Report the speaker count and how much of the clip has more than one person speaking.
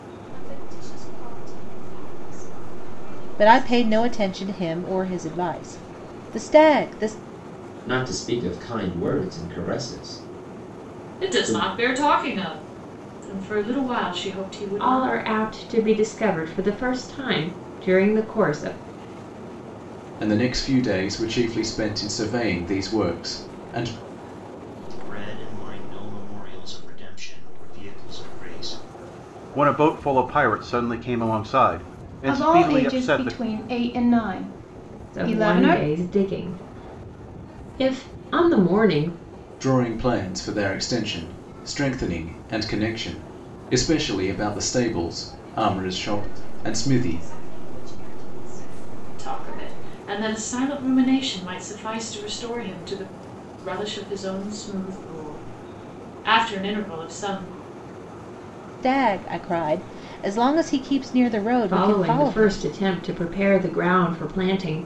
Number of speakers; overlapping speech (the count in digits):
9, about 10%